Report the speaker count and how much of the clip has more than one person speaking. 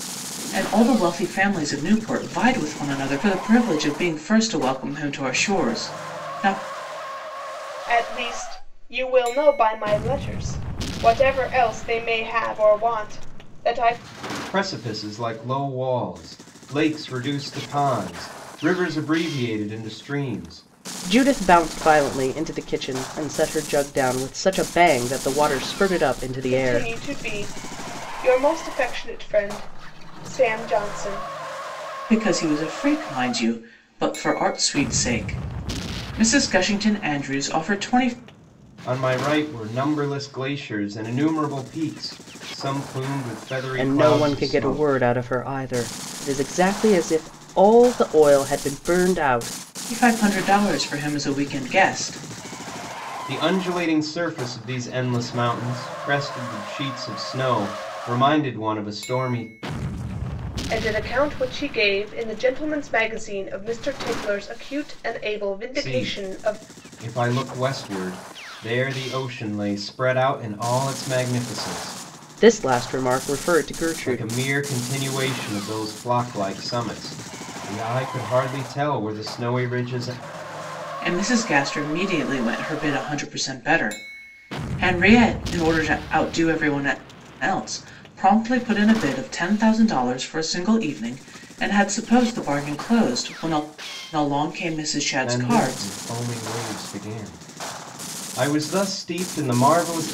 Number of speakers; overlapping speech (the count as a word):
four, about 4%